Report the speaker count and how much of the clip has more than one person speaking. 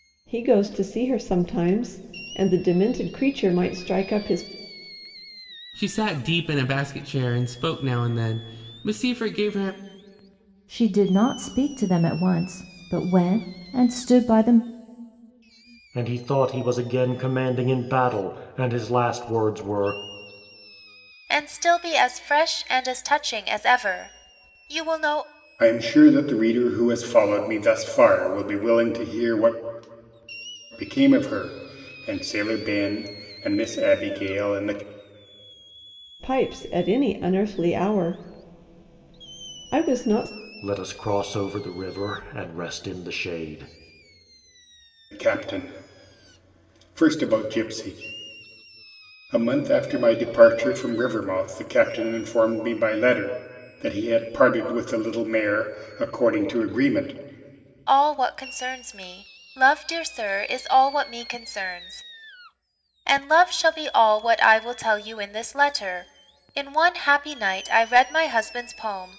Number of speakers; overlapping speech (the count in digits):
6, no overlap